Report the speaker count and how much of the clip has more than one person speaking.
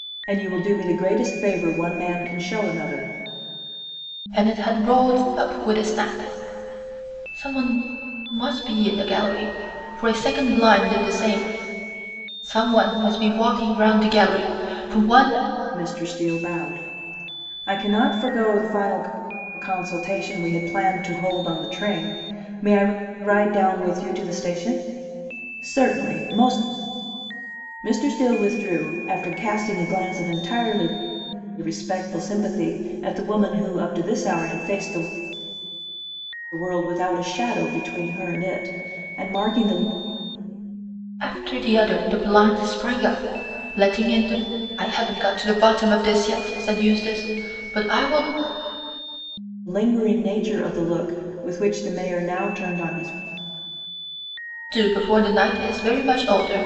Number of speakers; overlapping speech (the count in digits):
2, no overlap